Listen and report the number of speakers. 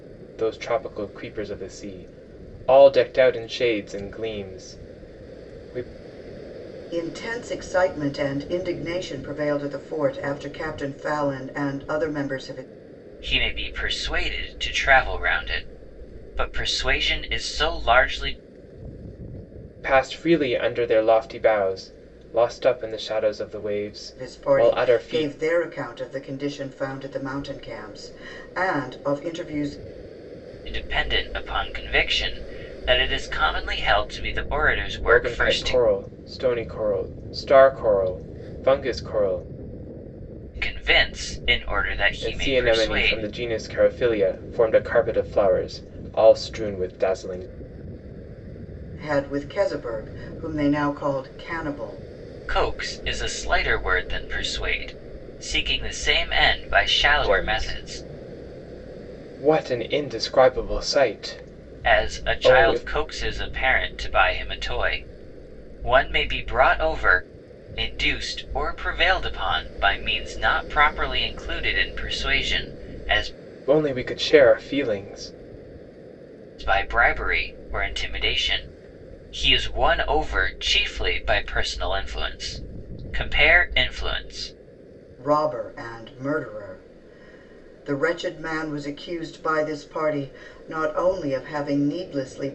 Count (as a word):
three